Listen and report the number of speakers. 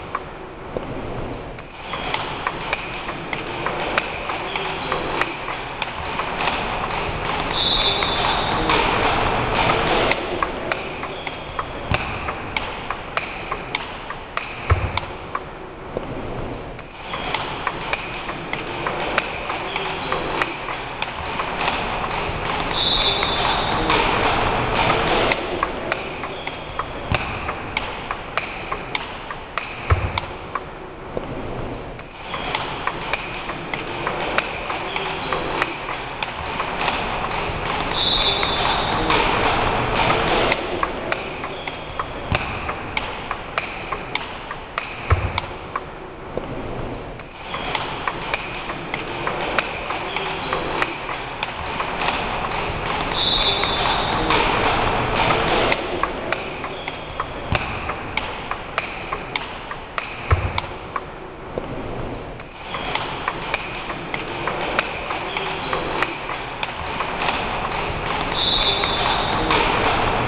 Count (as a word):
zero